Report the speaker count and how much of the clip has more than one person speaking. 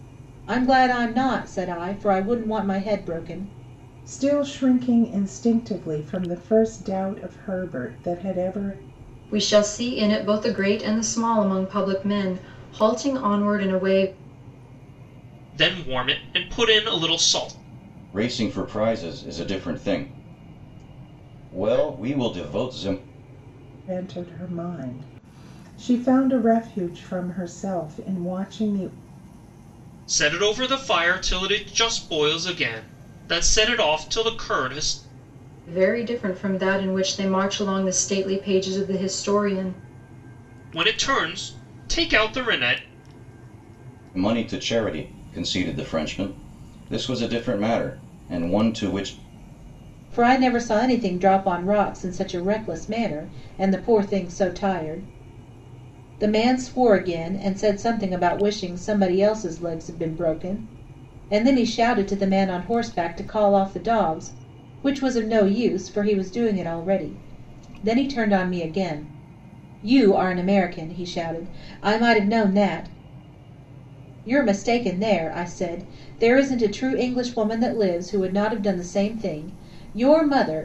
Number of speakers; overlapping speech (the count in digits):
5, no overlap